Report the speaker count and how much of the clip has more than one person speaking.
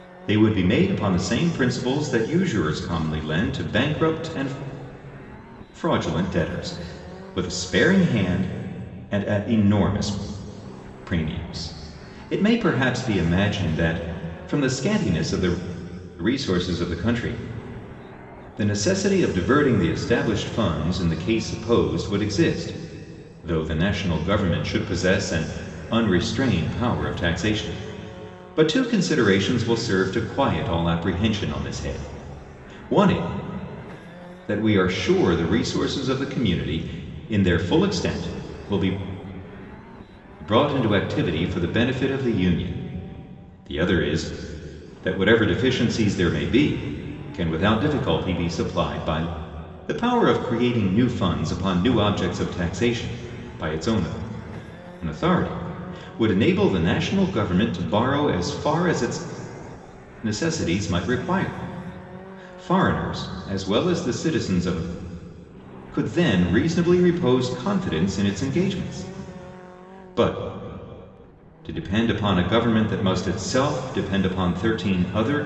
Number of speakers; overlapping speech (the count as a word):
one, no overlap